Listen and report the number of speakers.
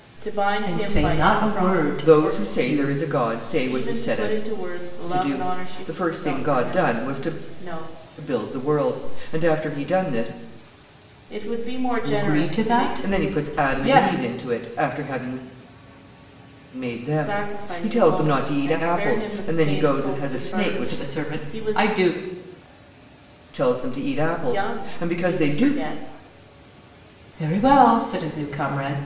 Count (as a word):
three